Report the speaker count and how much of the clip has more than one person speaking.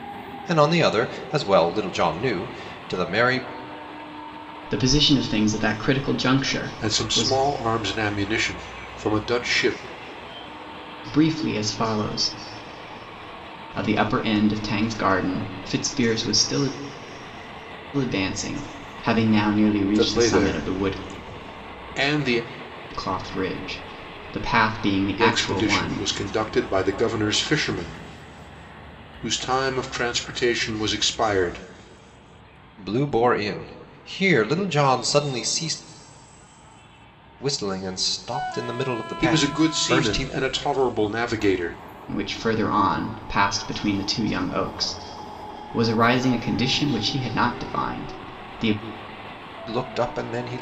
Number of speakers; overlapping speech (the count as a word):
three, about 7%